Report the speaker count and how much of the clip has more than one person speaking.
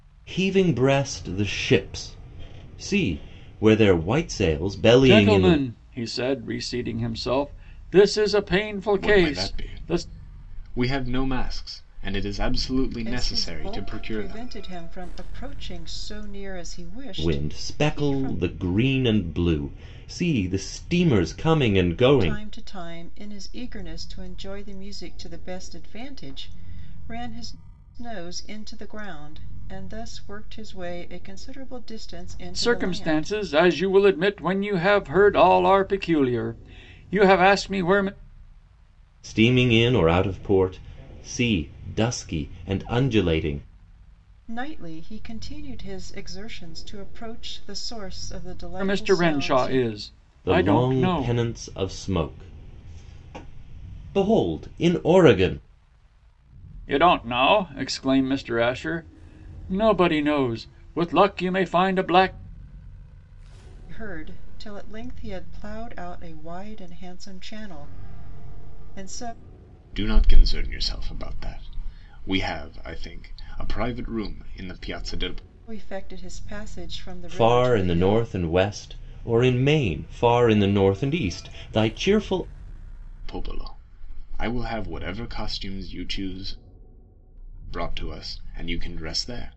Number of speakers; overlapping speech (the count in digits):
4, about 10%